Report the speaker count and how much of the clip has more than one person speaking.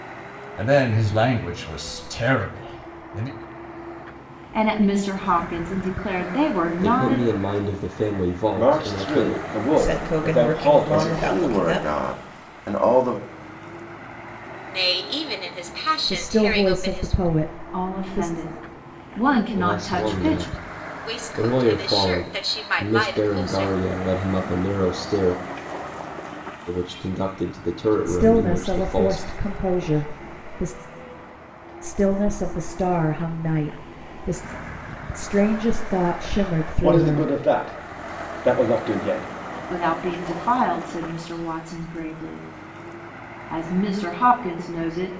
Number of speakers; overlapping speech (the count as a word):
eight, about 23%